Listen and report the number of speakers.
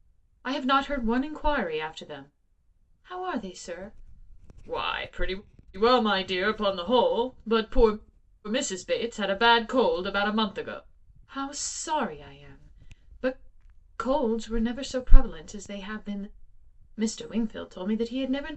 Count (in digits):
1